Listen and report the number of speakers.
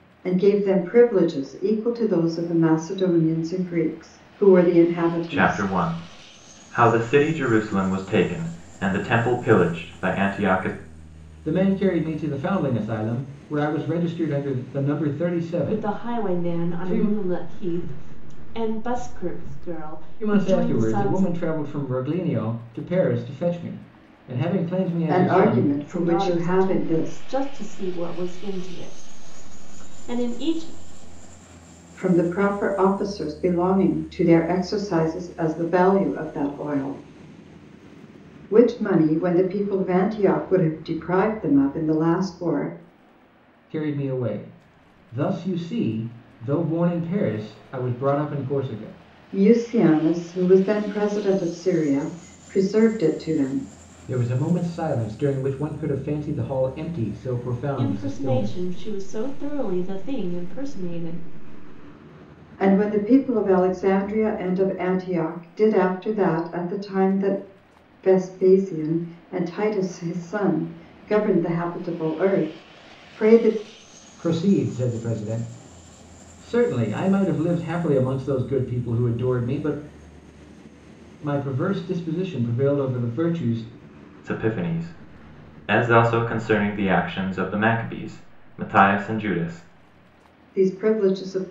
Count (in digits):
4